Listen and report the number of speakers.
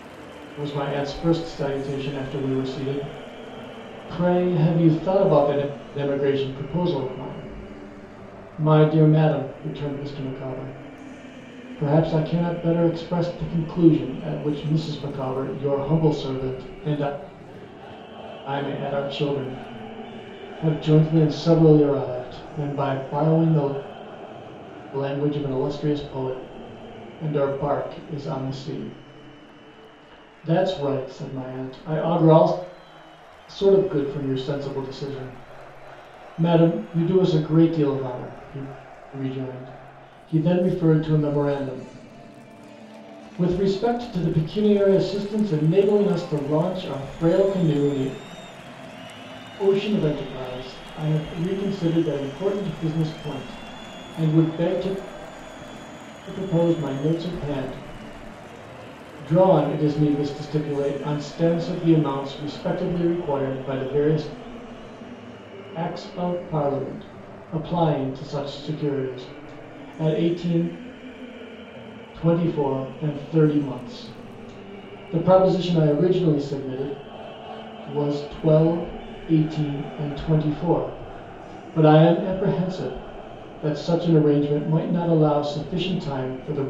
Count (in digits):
1